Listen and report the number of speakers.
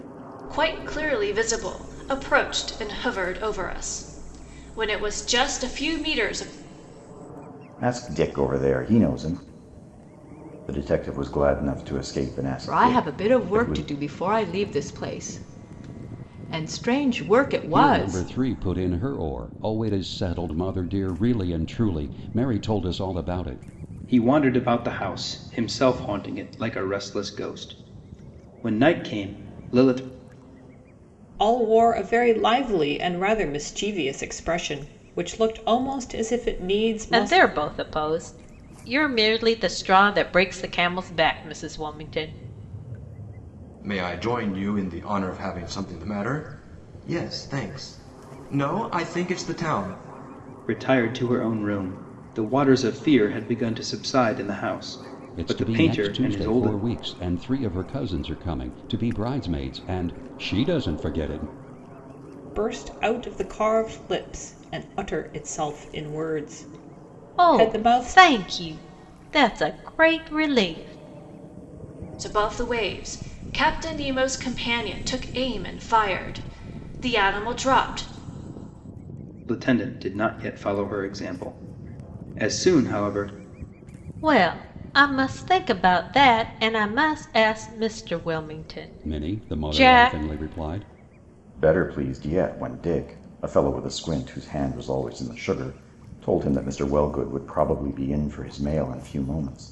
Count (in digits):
8